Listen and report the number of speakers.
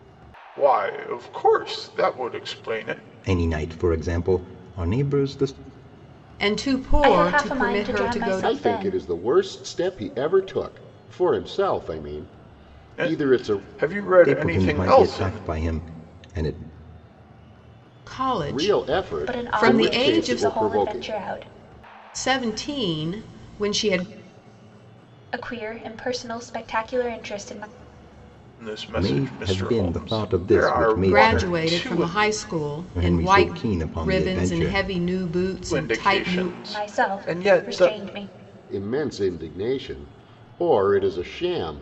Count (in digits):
5